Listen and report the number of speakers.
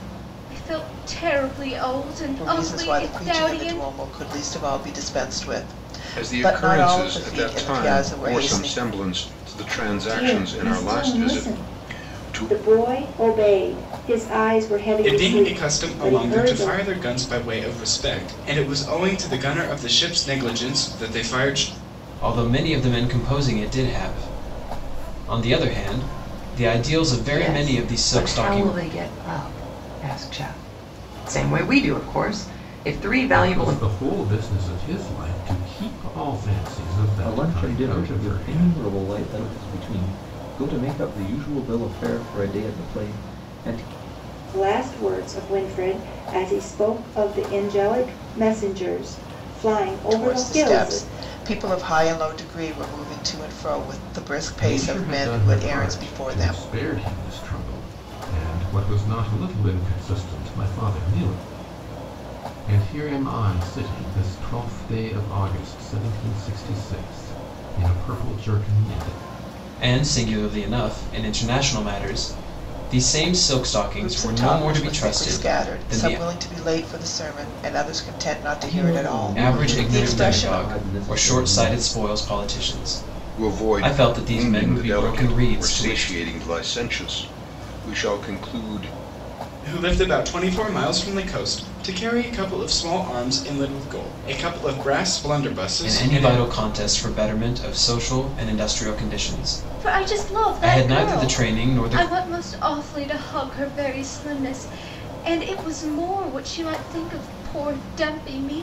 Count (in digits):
9